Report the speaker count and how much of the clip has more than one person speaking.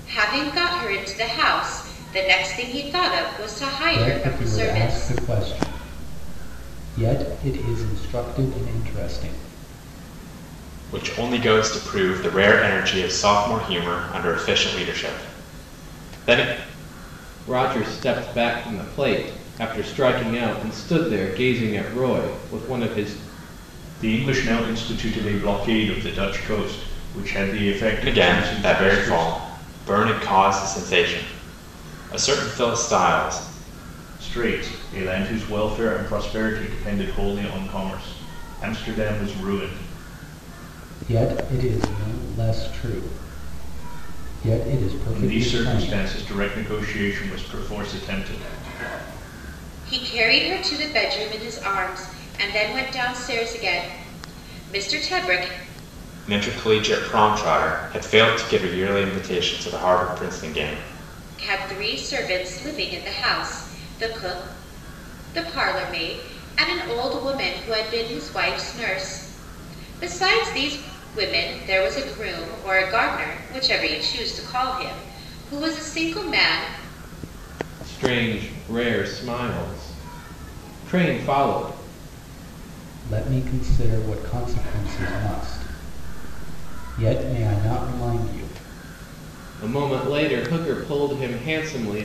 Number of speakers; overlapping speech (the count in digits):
5, about 4%